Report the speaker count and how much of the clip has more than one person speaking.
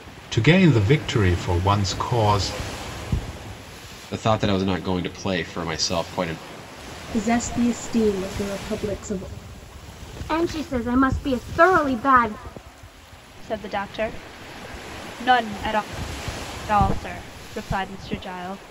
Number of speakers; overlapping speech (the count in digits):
5, no overlap